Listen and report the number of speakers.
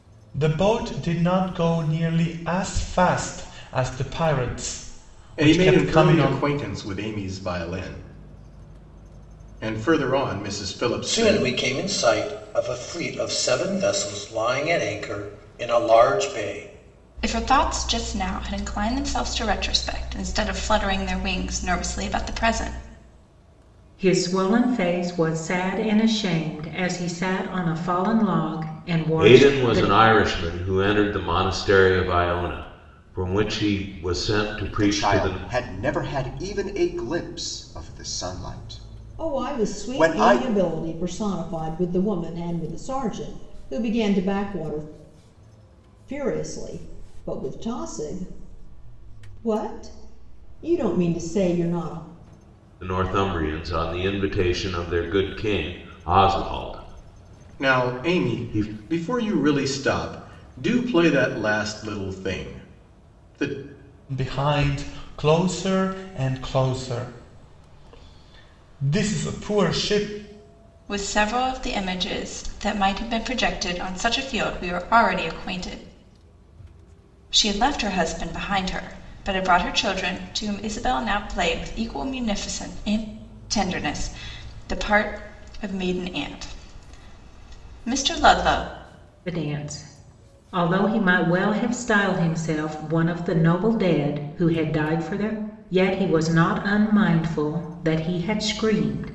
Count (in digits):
8